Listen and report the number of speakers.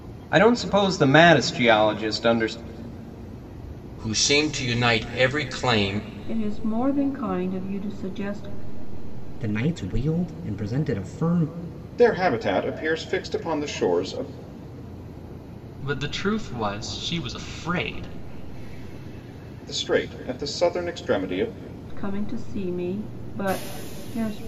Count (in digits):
6